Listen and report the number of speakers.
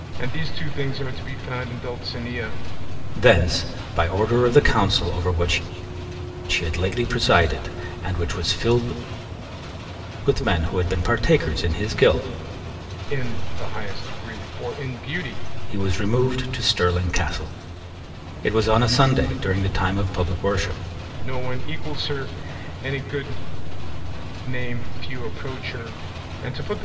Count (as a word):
two